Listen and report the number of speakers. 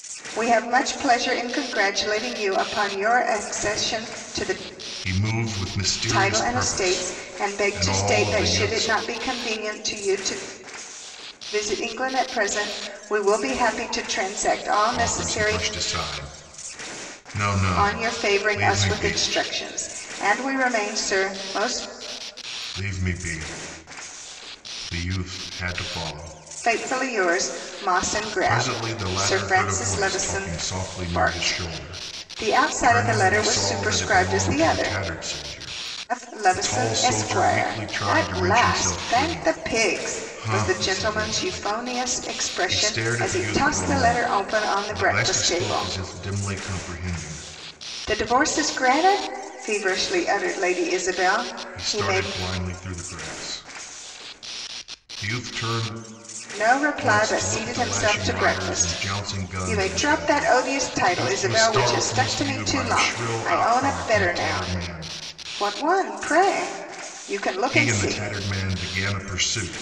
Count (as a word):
two